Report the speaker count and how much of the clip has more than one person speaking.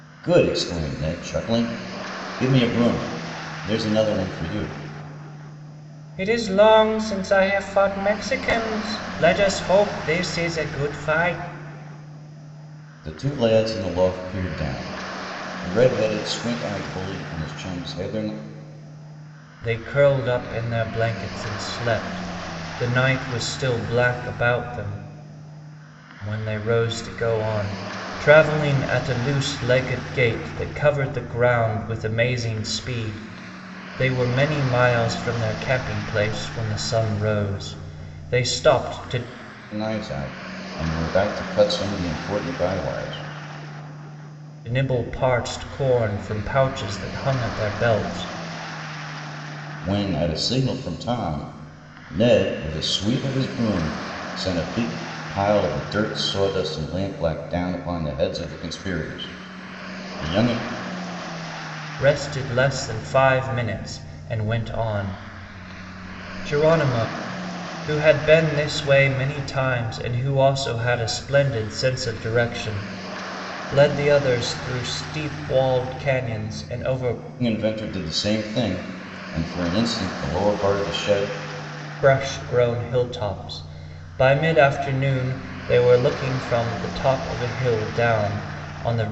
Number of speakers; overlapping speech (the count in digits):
2, no overlap